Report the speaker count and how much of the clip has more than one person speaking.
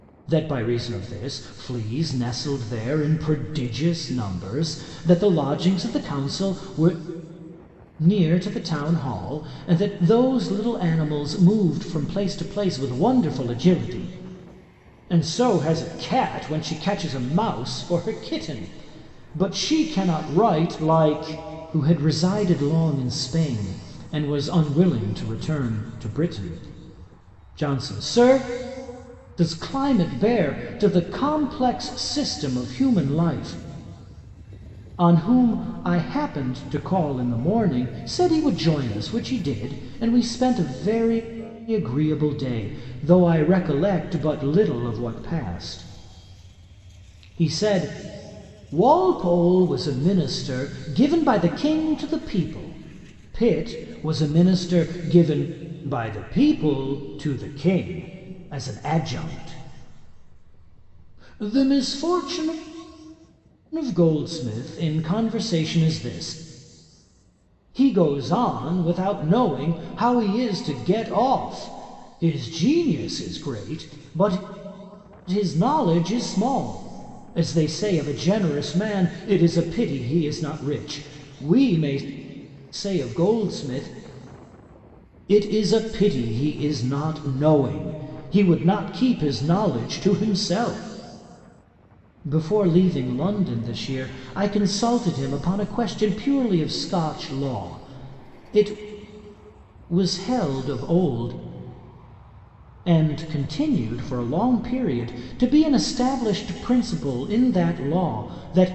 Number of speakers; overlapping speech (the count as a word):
one, no overlap